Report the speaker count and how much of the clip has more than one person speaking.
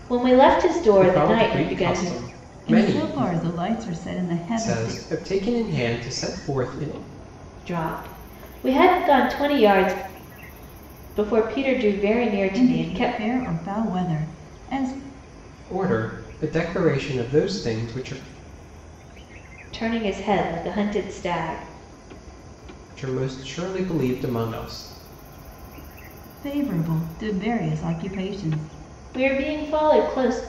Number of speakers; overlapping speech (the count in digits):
3, about 10%